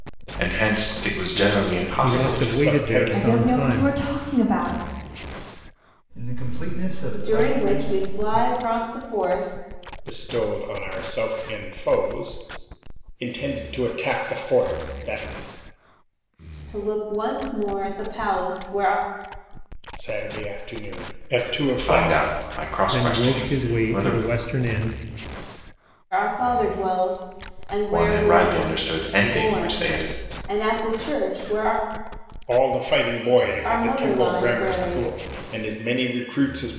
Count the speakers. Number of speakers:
6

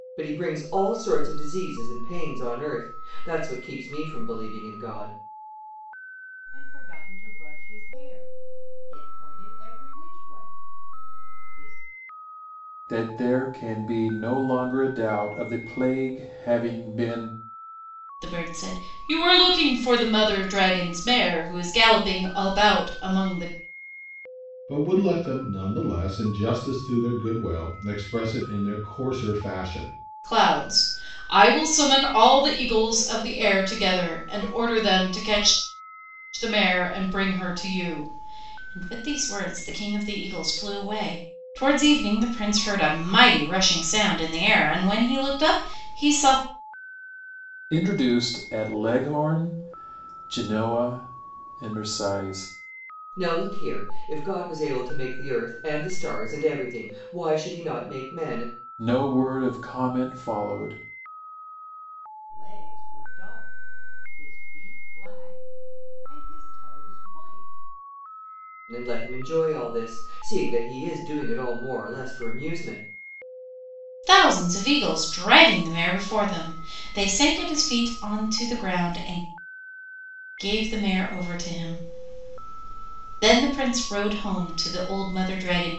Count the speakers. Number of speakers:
5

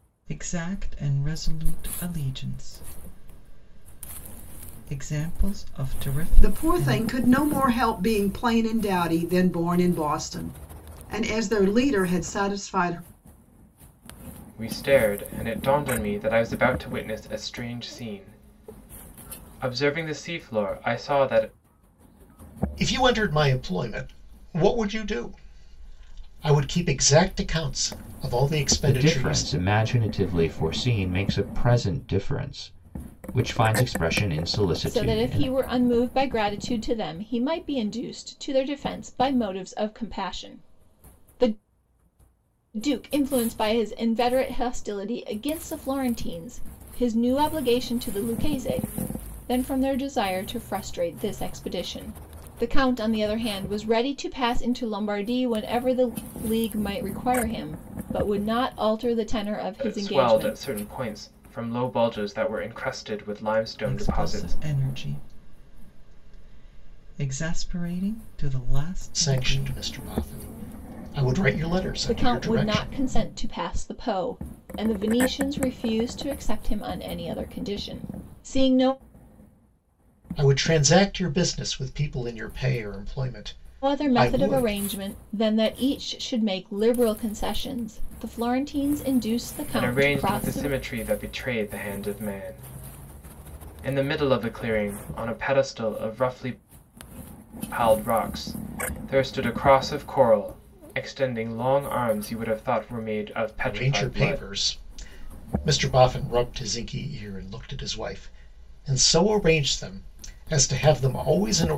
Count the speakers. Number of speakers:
6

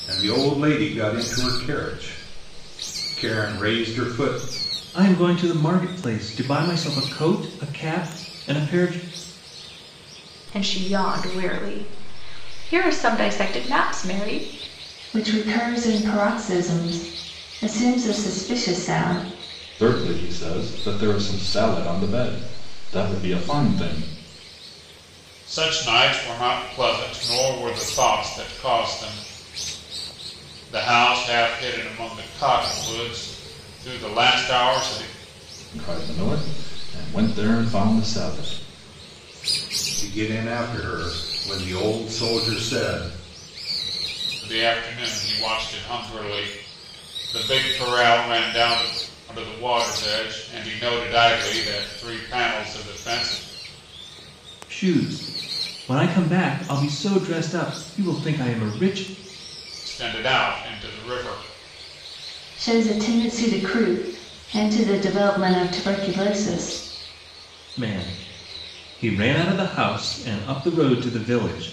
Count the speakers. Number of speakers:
6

